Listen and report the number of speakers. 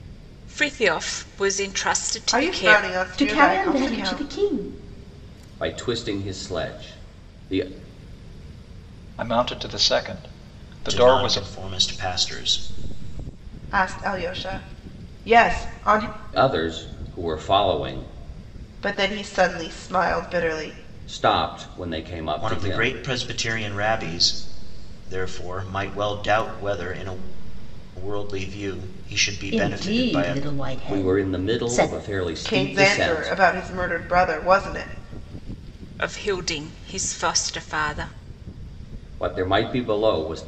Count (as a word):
six